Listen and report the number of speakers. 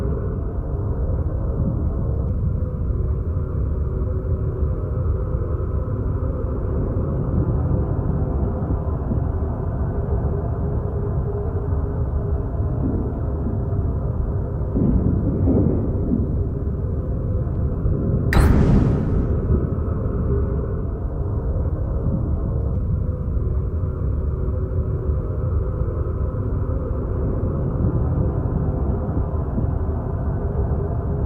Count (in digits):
0